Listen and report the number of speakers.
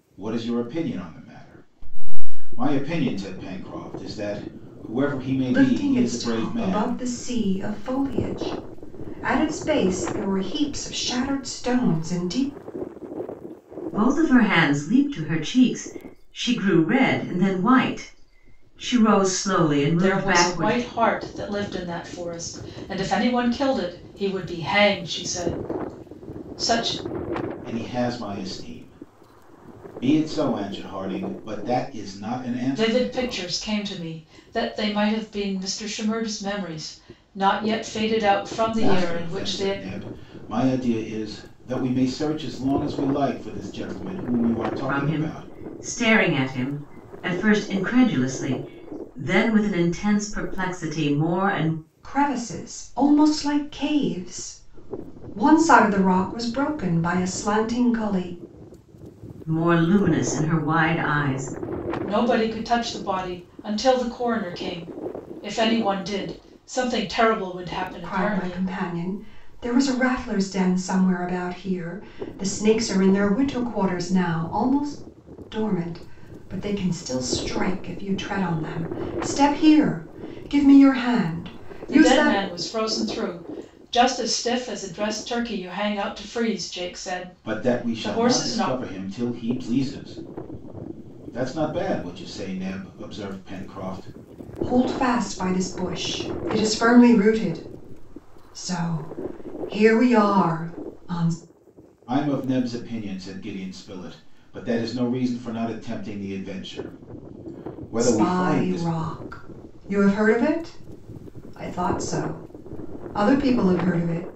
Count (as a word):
four